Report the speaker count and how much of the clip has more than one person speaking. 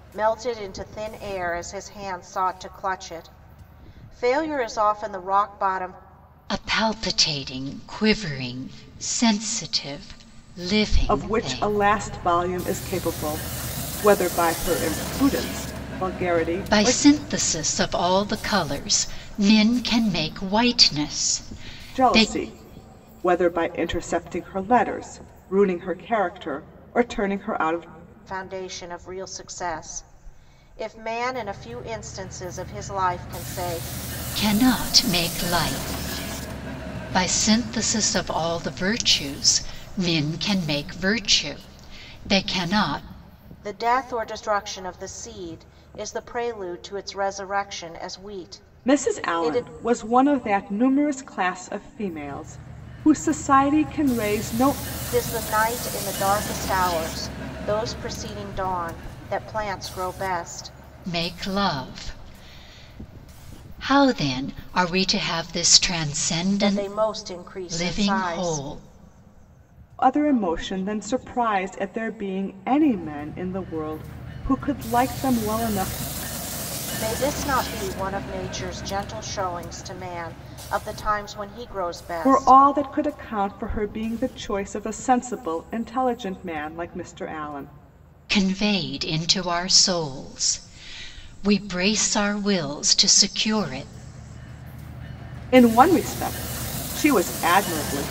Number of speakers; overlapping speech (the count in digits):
3, about 4%